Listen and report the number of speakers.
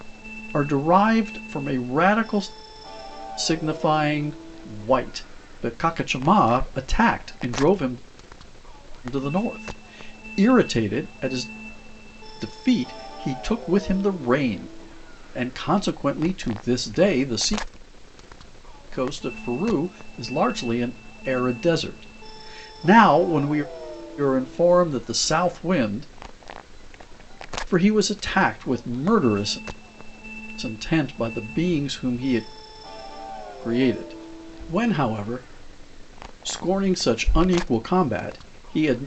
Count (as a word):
one